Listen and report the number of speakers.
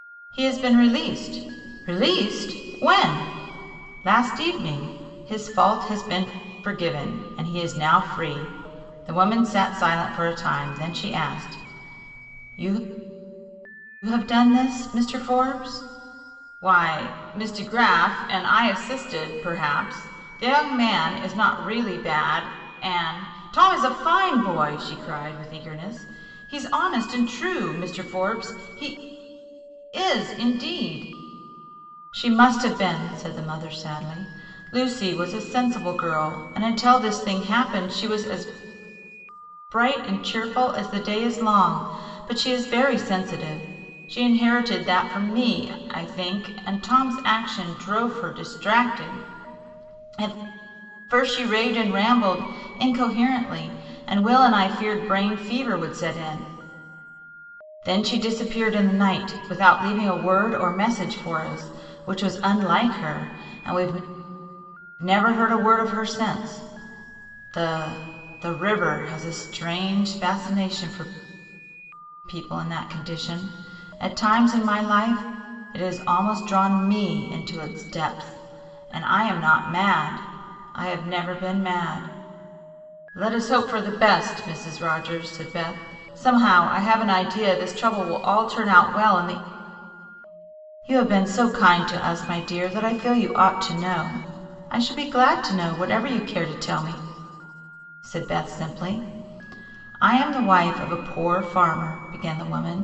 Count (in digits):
1